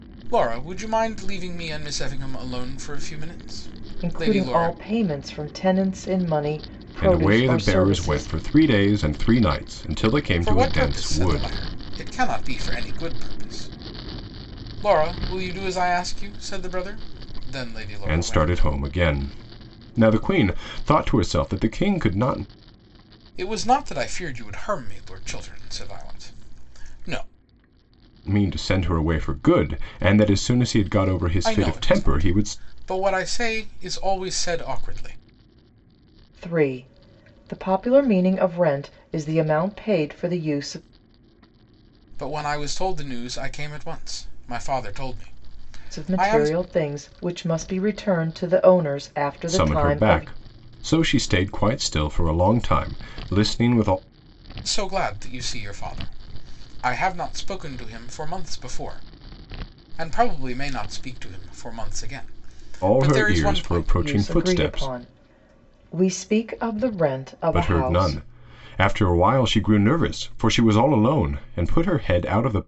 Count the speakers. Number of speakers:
three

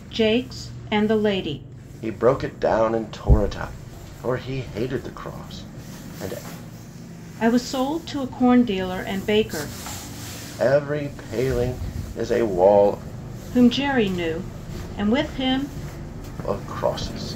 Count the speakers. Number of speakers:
two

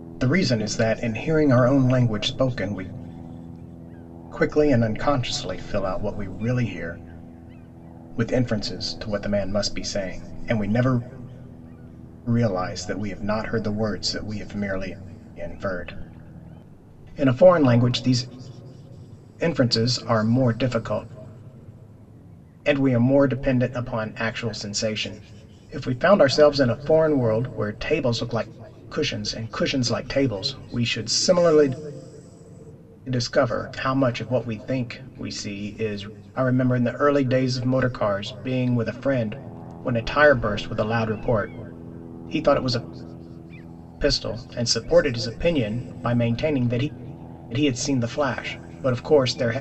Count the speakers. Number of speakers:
one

